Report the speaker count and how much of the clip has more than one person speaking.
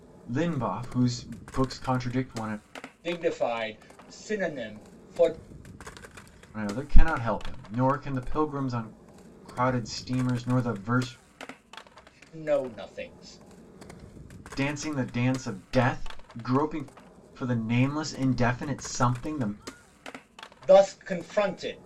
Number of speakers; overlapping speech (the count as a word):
two, no overlap